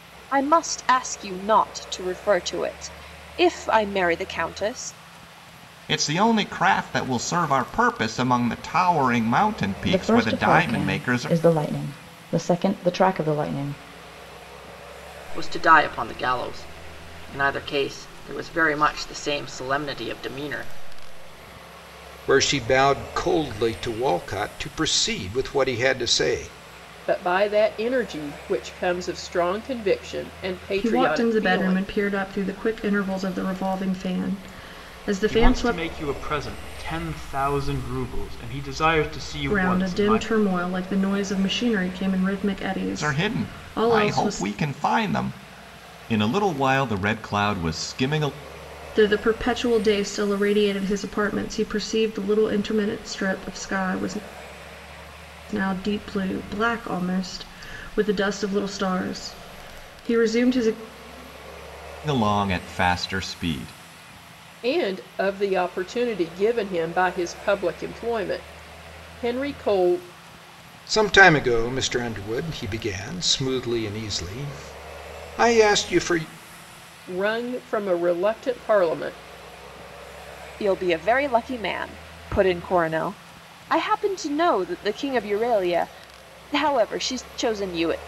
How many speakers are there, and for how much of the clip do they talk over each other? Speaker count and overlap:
eight, about 6%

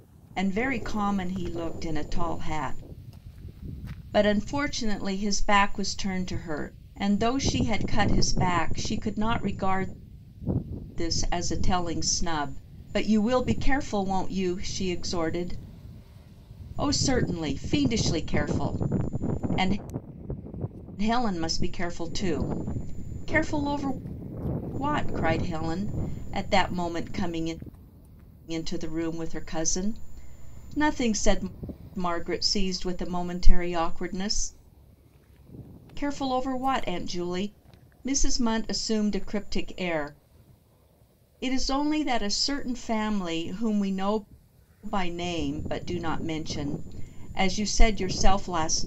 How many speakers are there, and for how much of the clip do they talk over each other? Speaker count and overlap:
one, no overlap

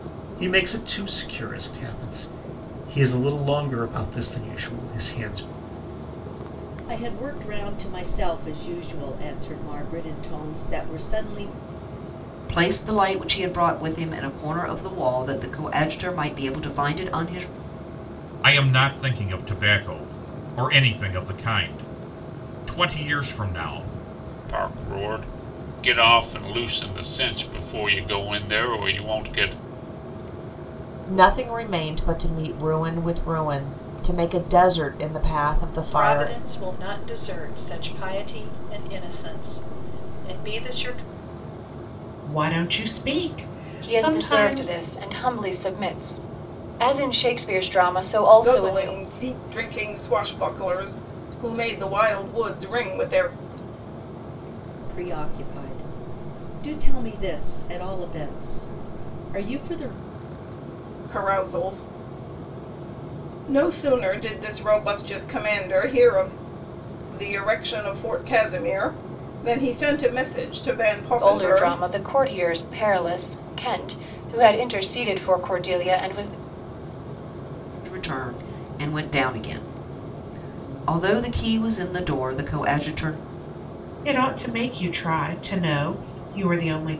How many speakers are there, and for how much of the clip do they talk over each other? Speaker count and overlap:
ten, about 3%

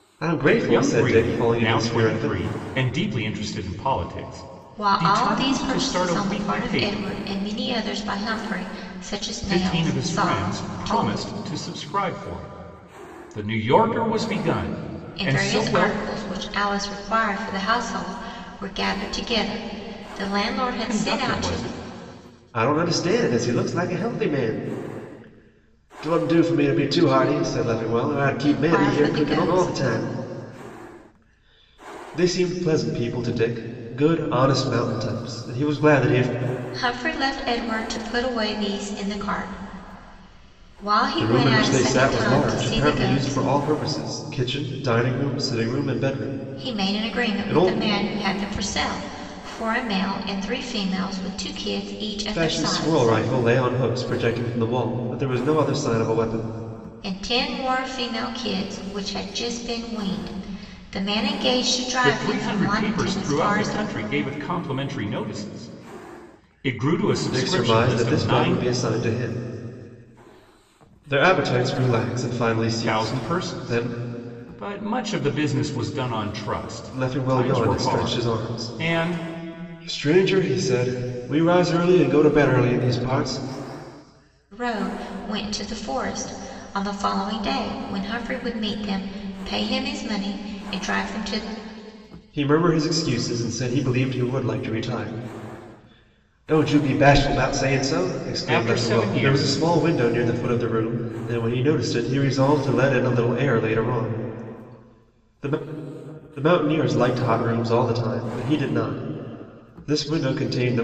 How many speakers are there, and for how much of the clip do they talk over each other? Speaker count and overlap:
three, about 19%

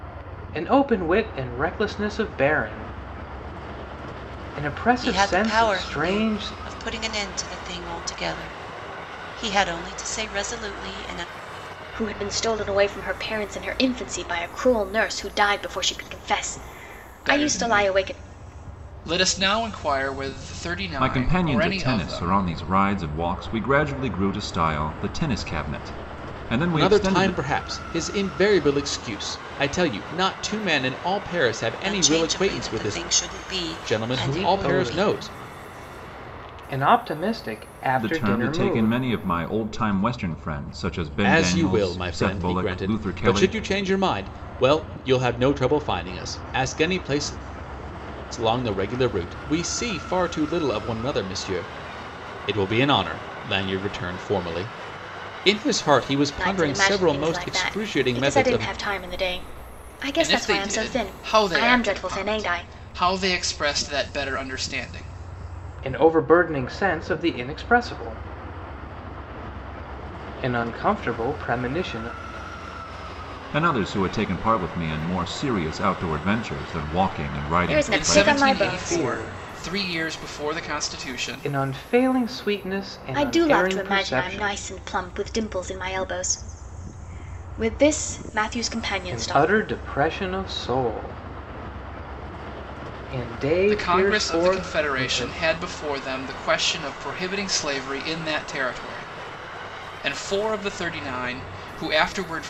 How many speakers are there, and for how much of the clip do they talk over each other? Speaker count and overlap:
six, about 23%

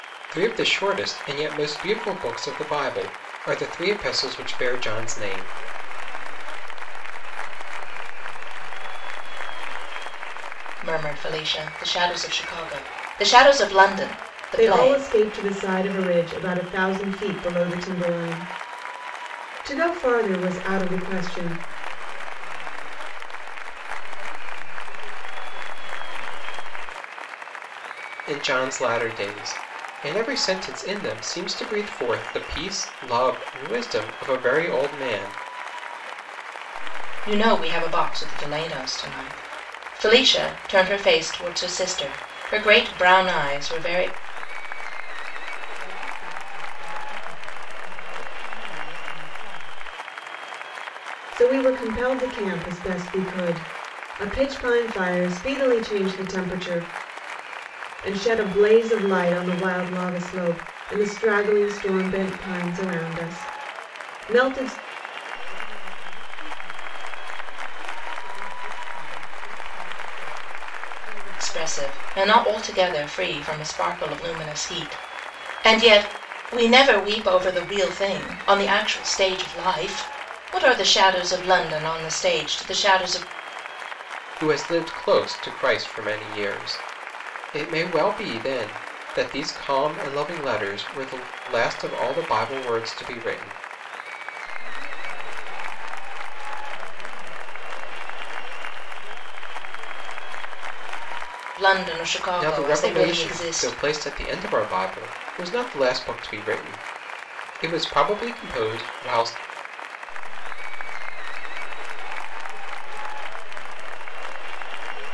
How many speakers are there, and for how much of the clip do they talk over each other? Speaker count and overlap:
four, about 7%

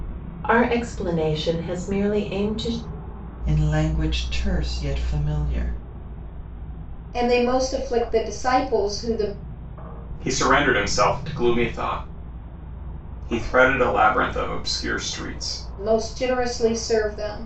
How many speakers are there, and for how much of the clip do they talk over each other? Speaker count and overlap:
four, no overlap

